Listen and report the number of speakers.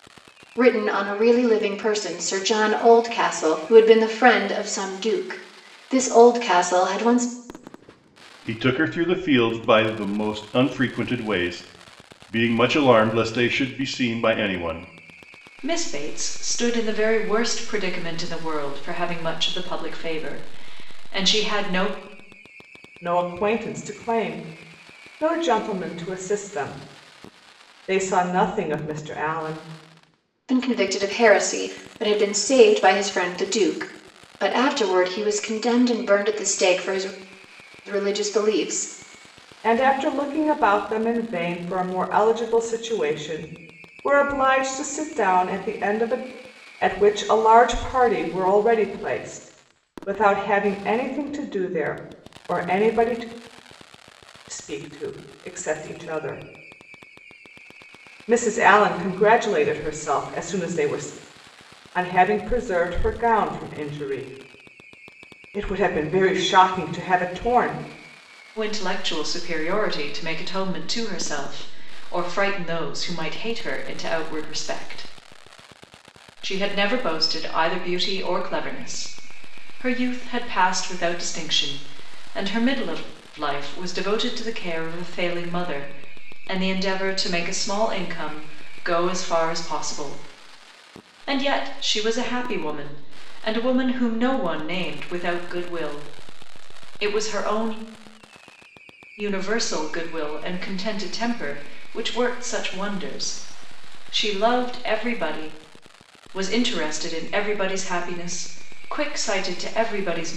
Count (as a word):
four